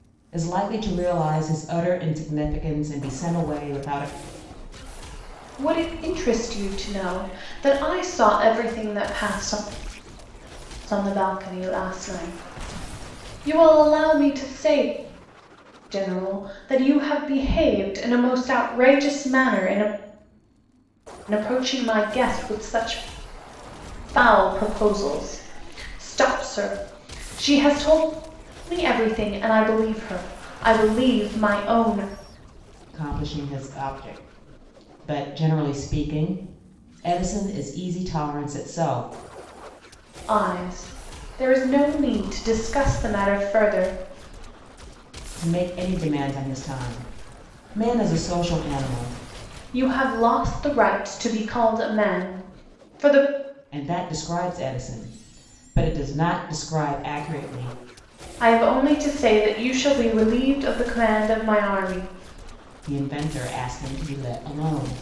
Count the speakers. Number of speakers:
two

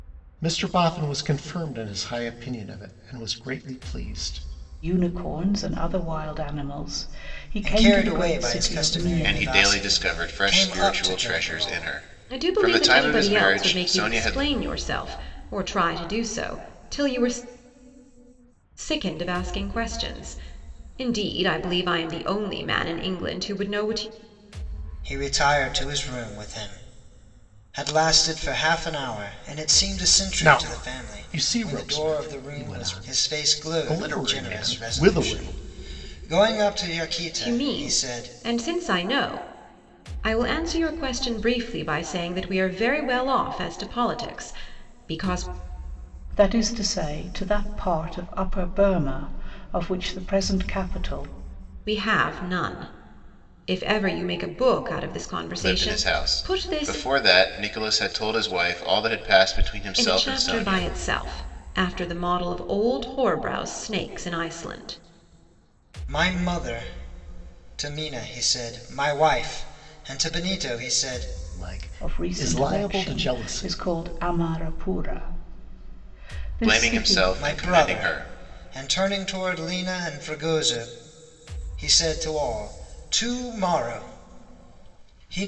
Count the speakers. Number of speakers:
five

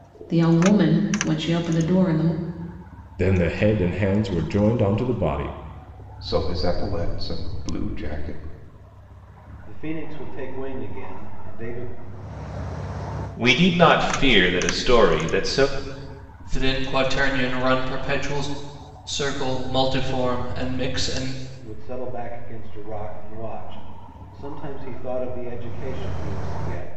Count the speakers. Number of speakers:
six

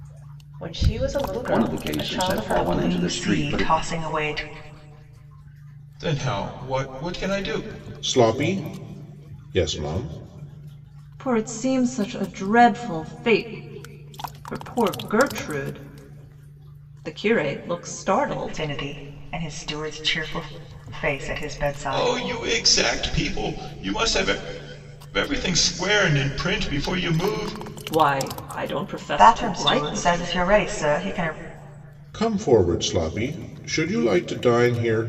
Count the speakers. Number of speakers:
six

